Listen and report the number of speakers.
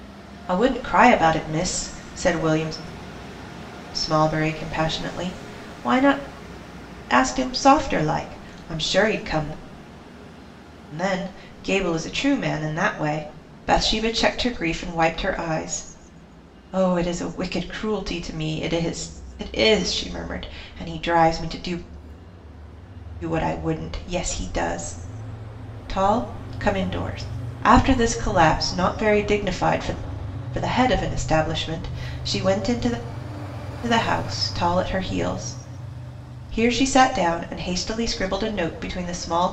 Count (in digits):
1